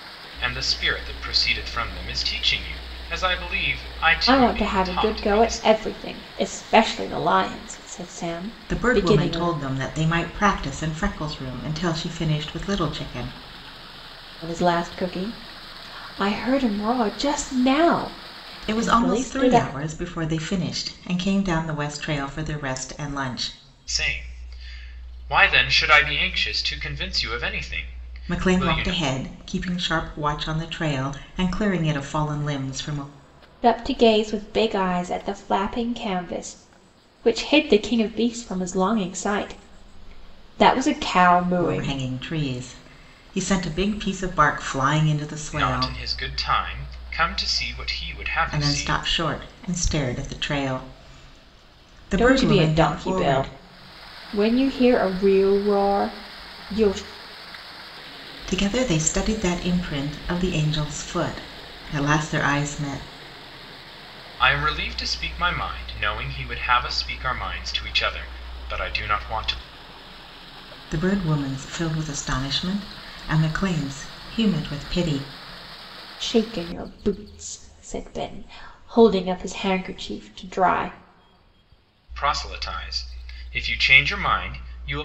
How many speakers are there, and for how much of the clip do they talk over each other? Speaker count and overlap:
3, about 8%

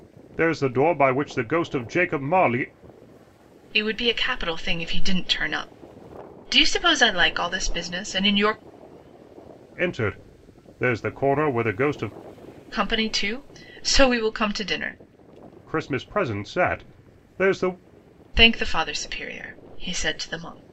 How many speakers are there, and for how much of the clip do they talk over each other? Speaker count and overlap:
2, no overlap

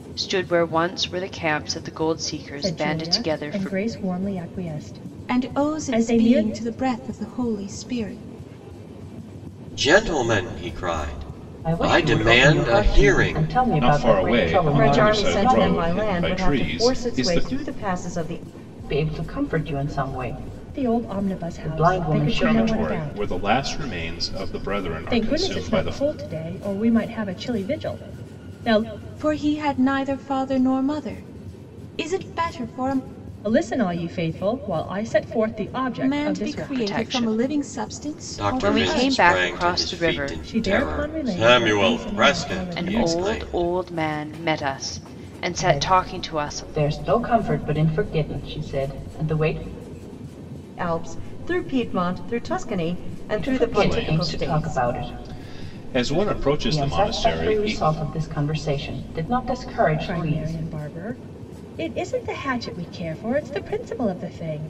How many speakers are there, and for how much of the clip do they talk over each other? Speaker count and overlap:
7, about 37%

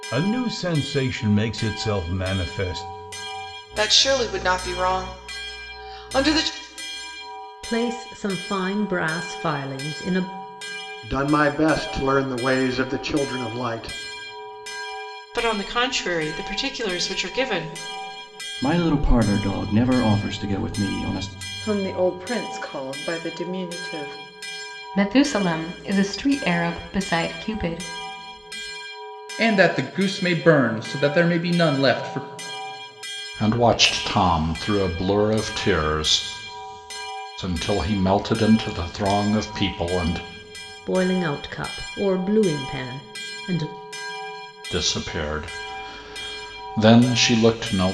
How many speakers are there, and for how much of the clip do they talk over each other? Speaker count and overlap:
10, no overlap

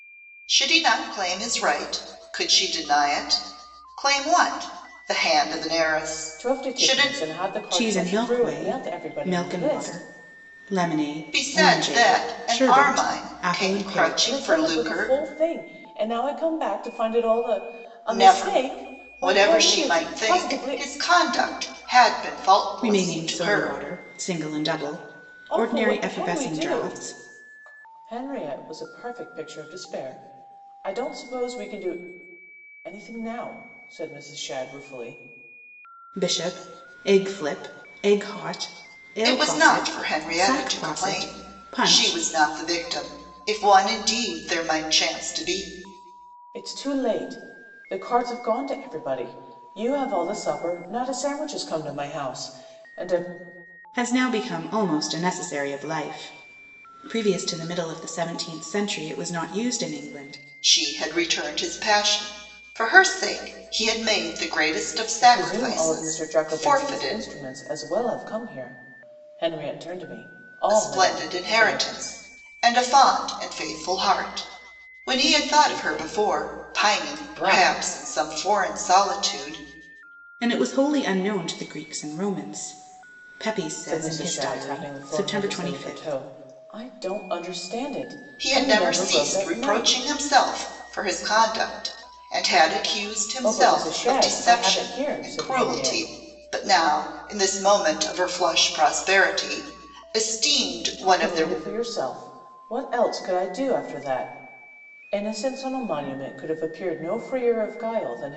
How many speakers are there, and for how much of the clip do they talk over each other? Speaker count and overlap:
3, about 26%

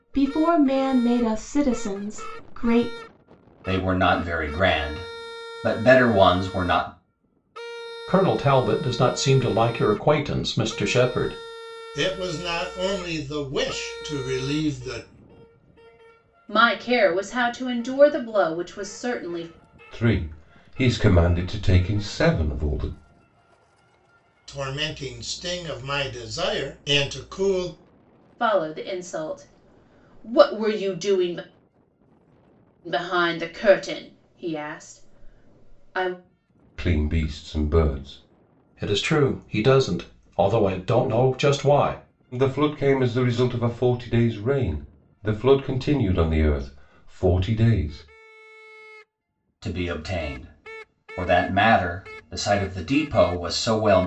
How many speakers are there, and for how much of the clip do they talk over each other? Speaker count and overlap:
6, no overlap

